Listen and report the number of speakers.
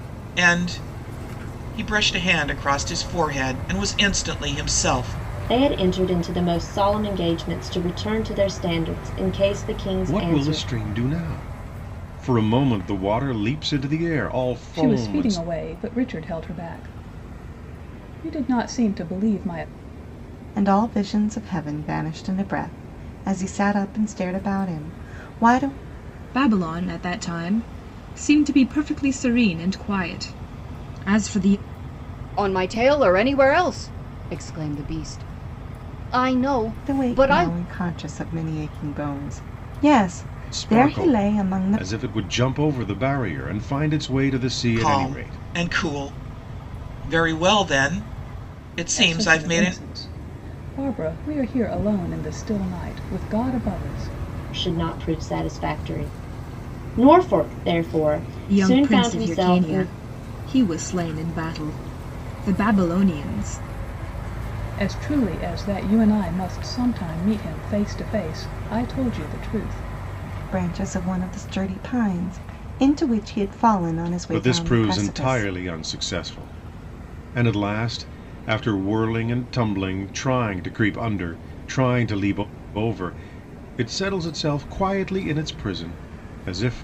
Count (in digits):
7